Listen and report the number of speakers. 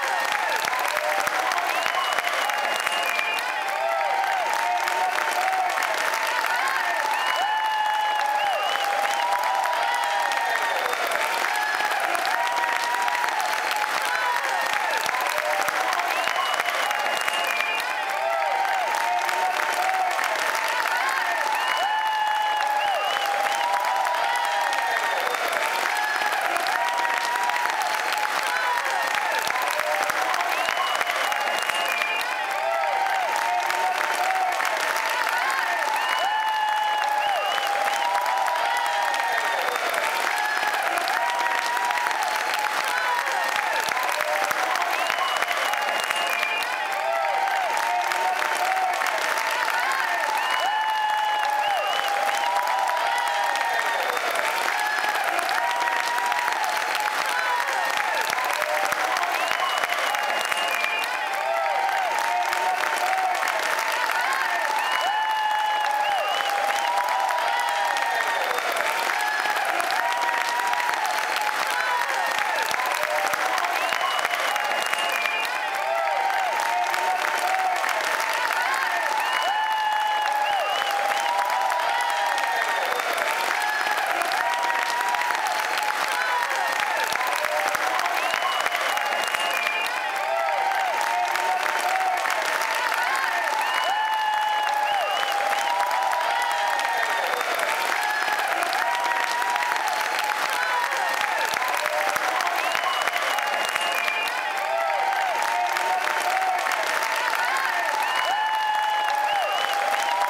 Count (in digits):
0